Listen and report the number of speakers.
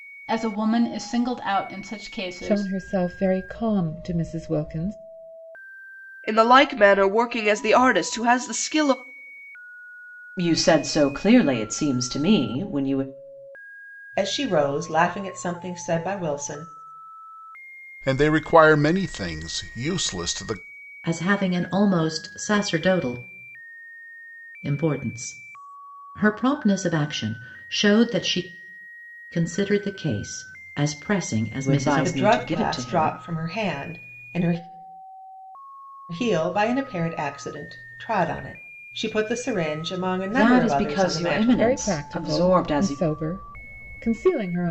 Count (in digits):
7